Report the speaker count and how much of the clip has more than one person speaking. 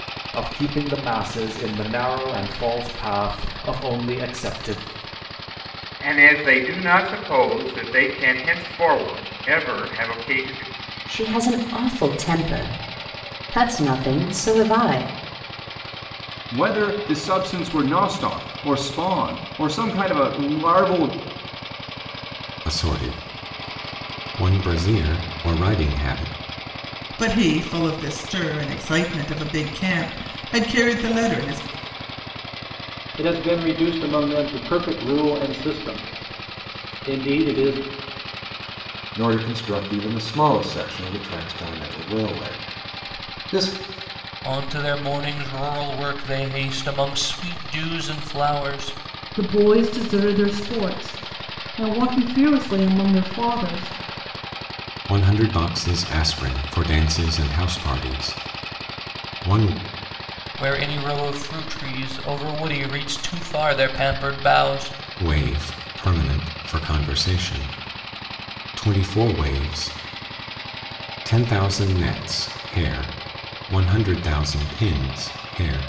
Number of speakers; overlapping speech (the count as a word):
ten, no overlap